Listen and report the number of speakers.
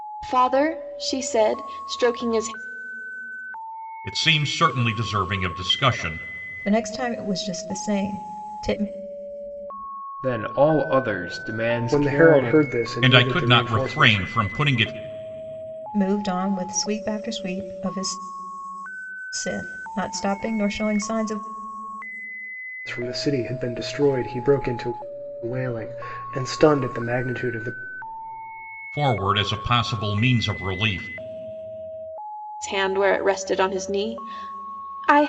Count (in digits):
5